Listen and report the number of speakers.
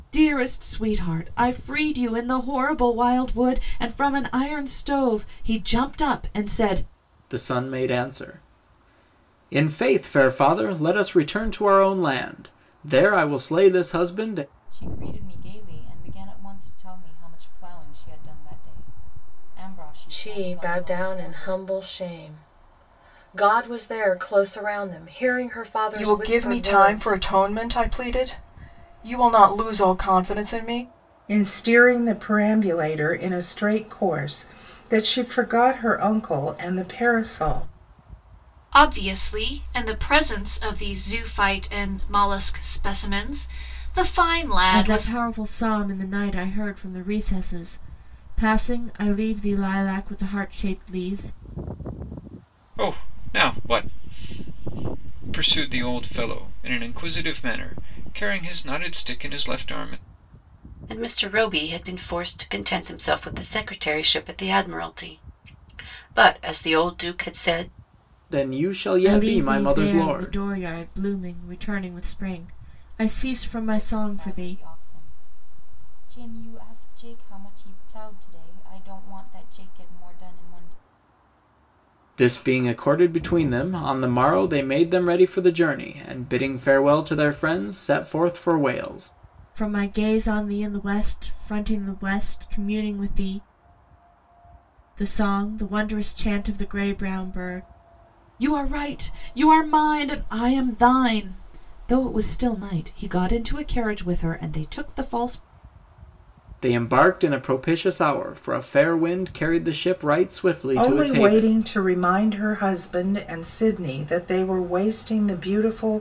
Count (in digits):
10